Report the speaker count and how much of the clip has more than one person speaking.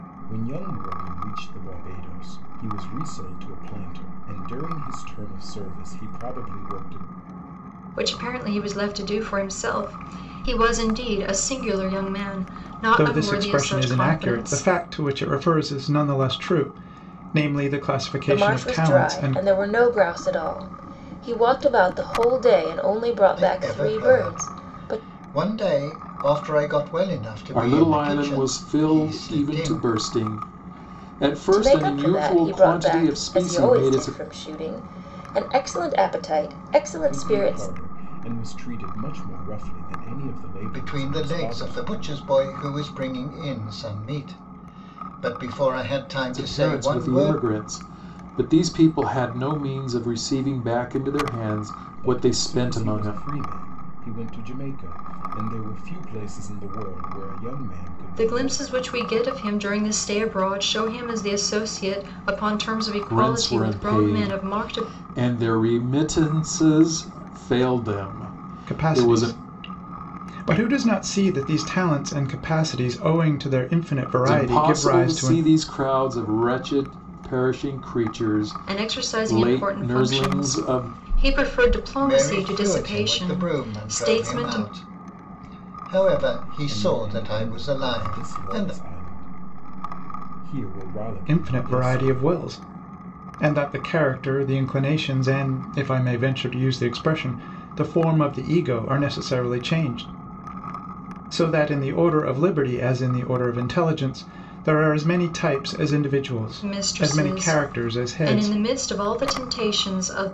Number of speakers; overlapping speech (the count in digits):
6, about 27%